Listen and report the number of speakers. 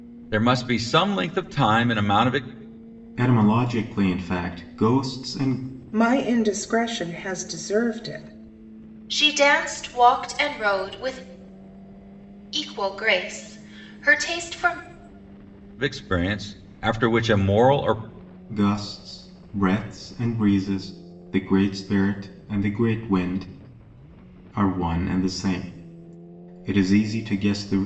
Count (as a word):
four